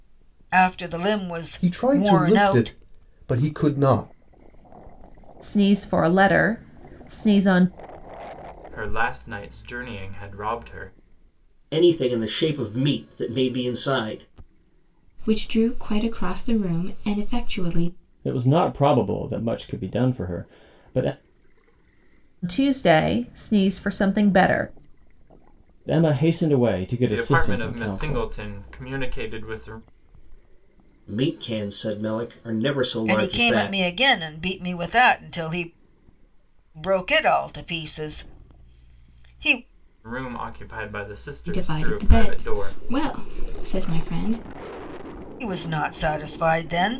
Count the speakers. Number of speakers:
7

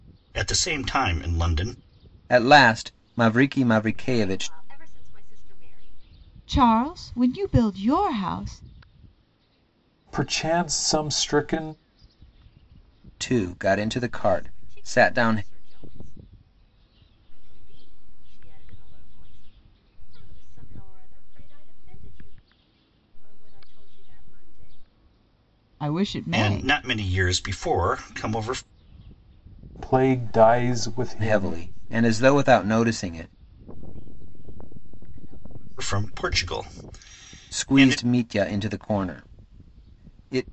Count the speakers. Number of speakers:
5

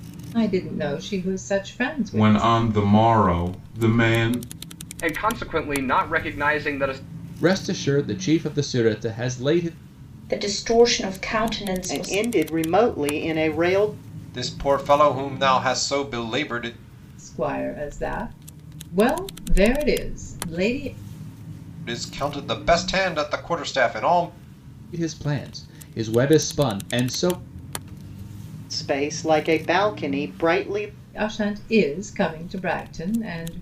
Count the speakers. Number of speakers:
7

